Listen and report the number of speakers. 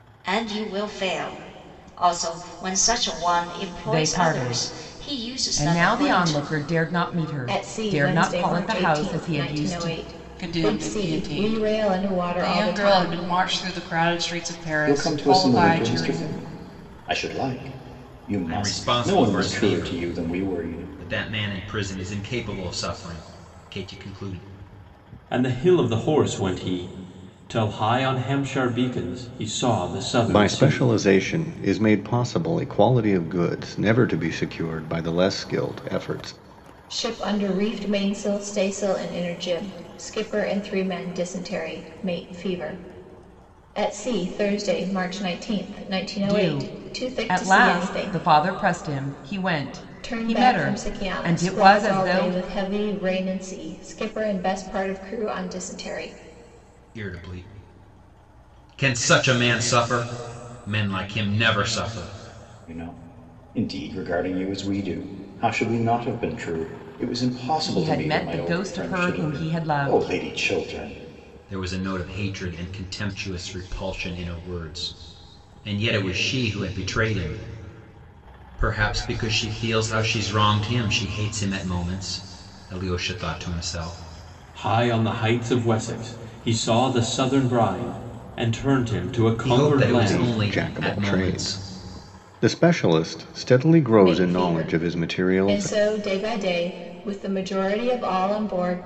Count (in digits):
8